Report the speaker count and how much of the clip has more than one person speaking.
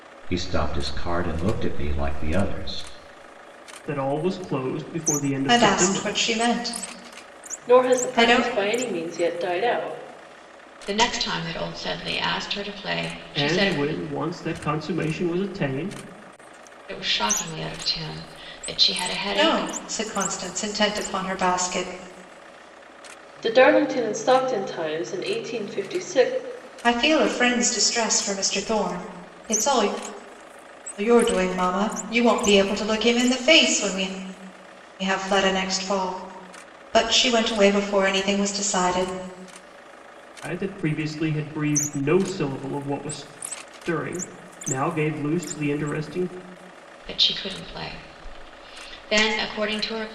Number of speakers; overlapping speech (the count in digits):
5, about 5%